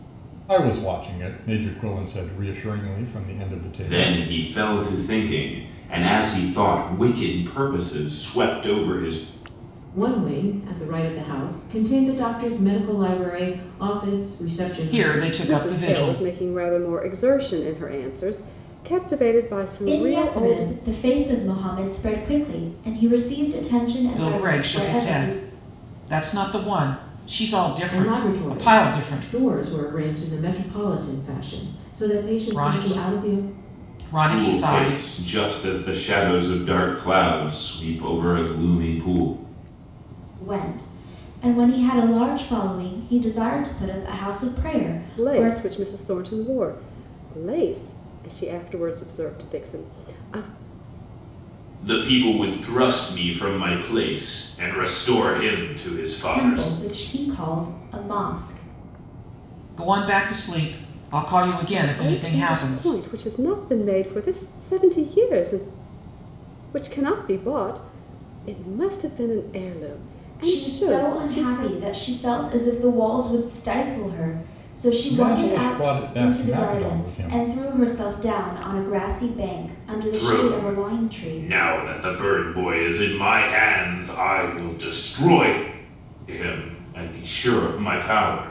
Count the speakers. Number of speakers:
six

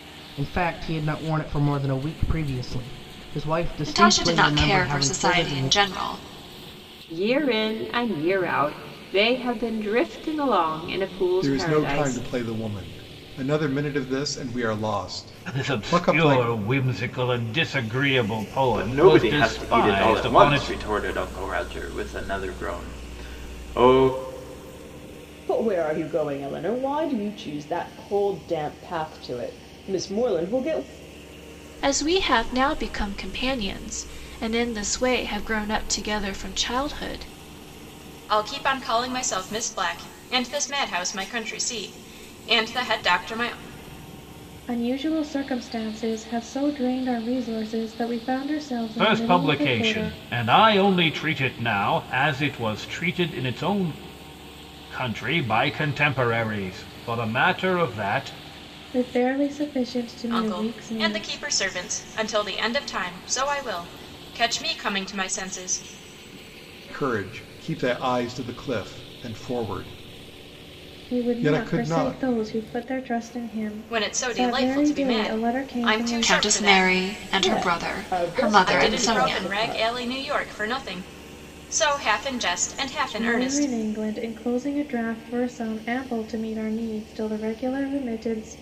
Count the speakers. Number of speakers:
ten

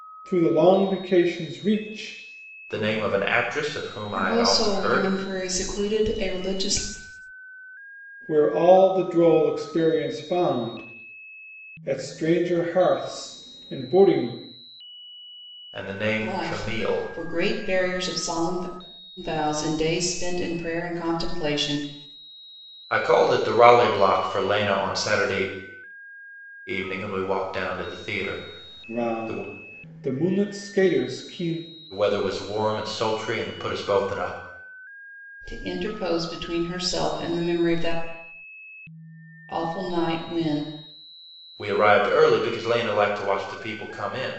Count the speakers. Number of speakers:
three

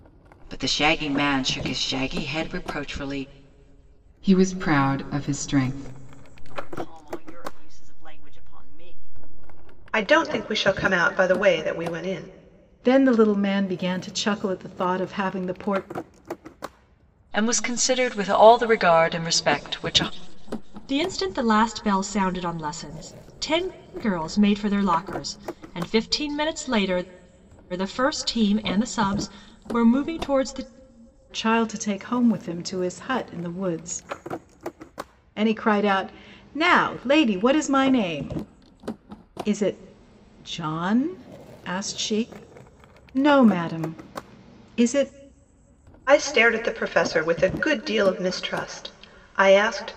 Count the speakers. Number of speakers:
seven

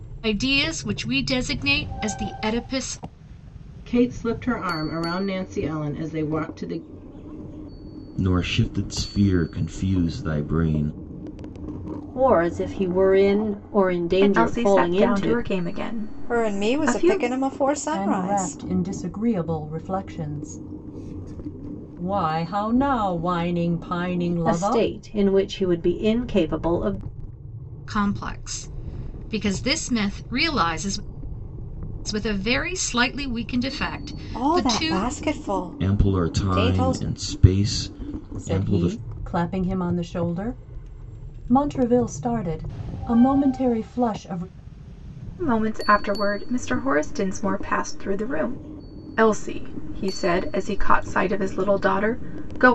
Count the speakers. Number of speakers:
seven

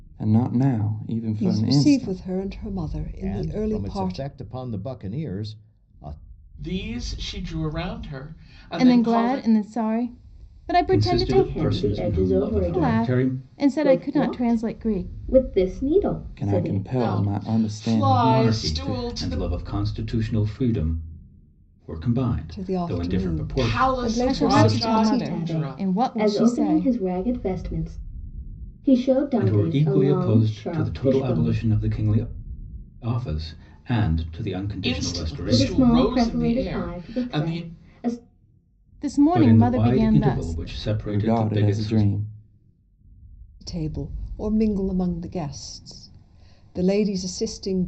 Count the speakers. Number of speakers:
seven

